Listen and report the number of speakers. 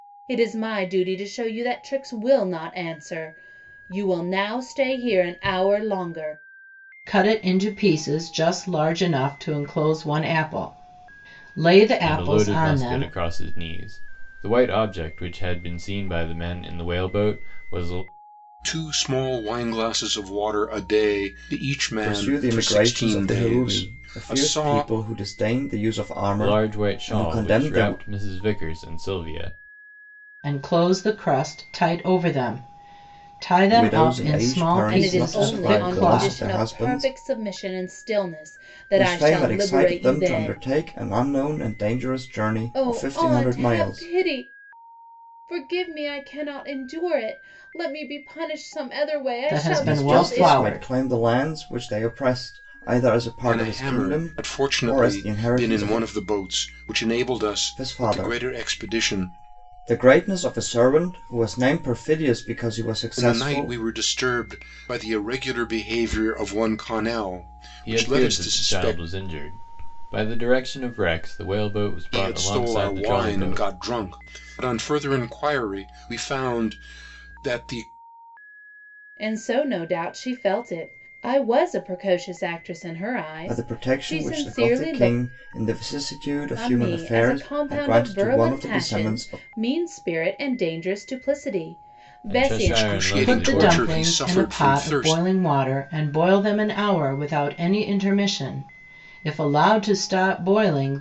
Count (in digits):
5